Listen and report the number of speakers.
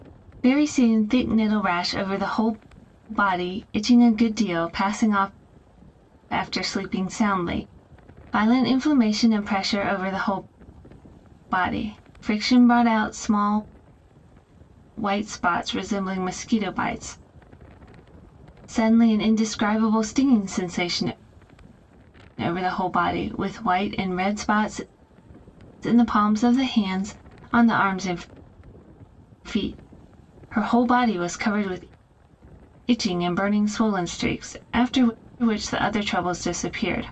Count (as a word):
one